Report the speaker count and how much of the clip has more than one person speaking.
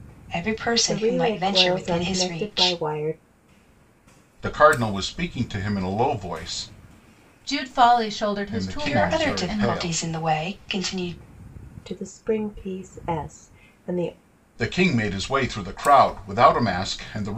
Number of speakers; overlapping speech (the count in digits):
4, about 20%